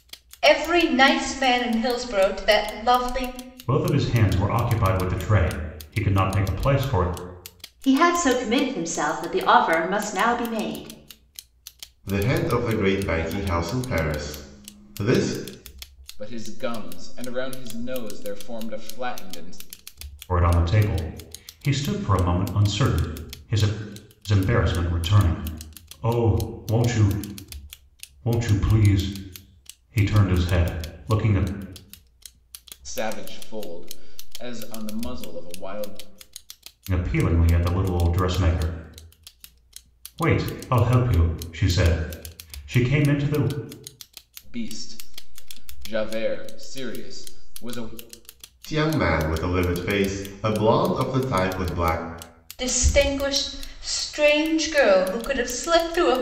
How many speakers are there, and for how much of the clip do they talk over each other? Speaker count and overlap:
five, no overlap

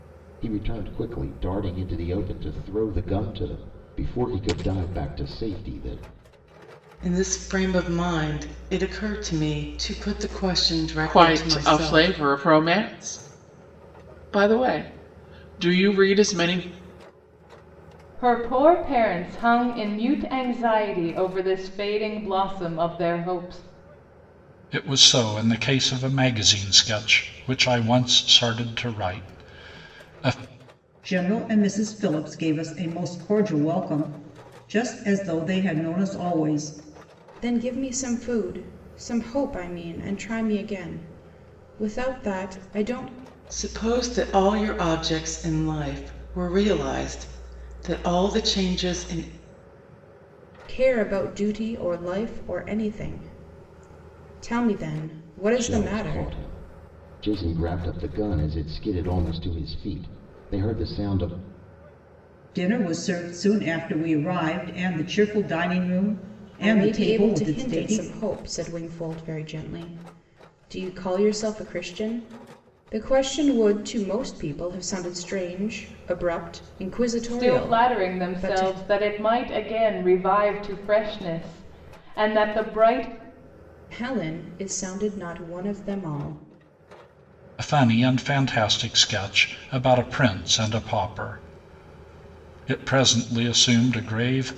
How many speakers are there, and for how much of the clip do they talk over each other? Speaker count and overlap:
seven, about 5%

